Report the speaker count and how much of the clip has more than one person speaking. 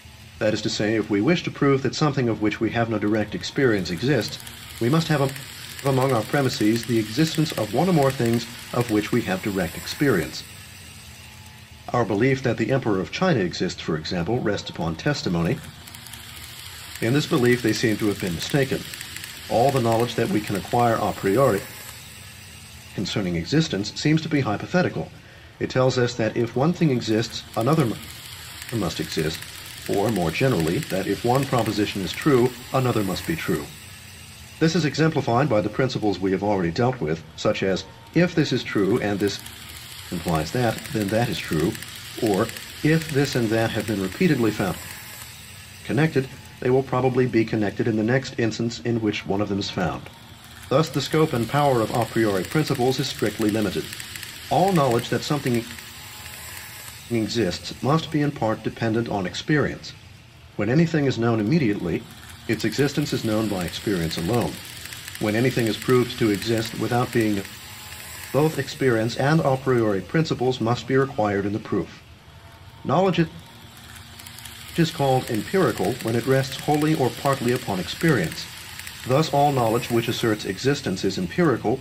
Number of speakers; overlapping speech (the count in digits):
1, no overlap